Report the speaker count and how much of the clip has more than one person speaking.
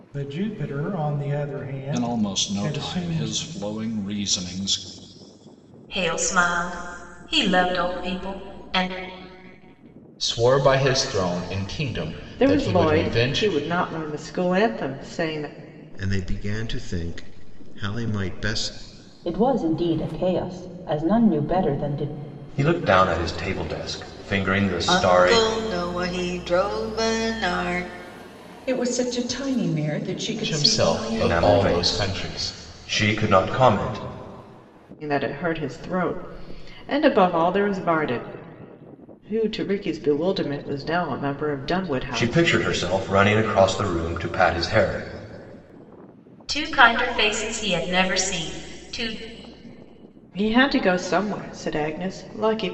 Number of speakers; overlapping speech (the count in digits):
10, about 11%